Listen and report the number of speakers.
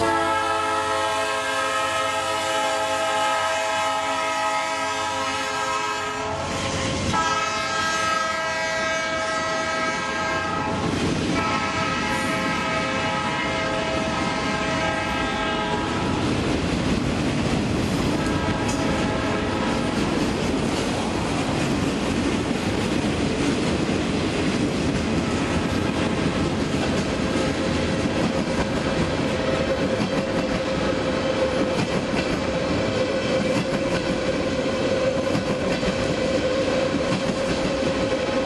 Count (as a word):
zero